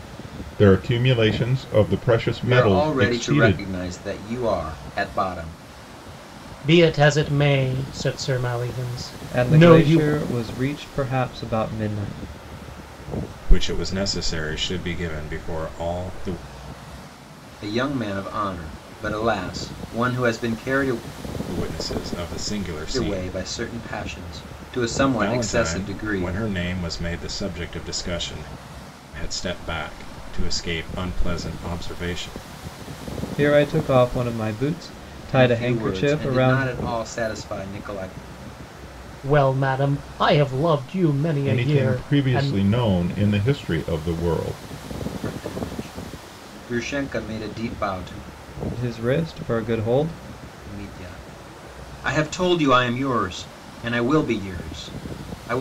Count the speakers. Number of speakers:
5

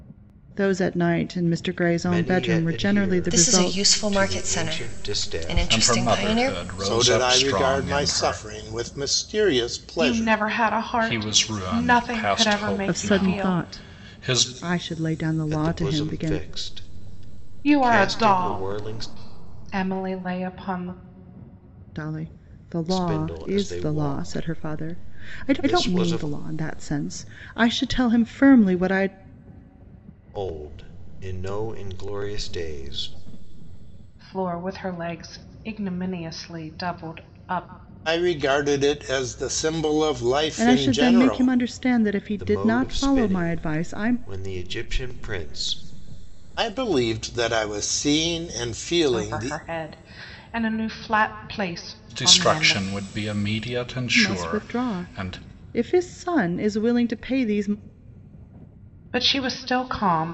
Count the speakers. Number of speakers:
6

